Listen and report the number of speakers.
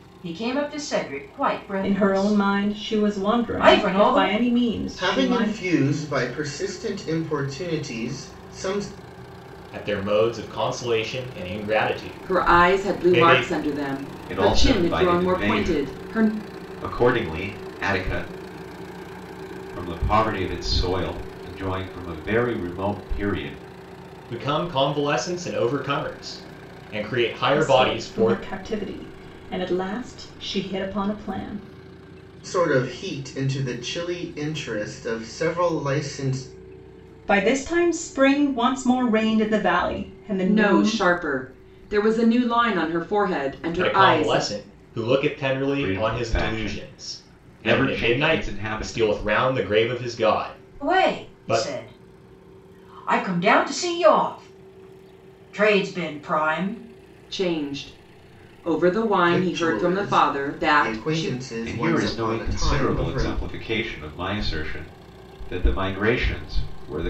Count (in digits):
6